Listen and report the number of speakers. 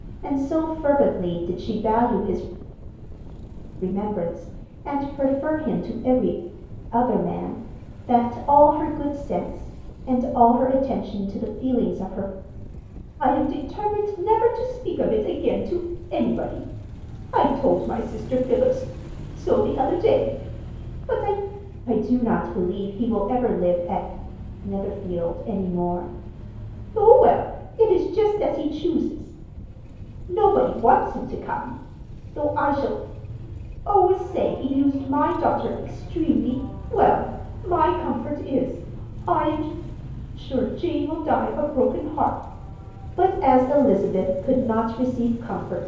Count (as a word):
one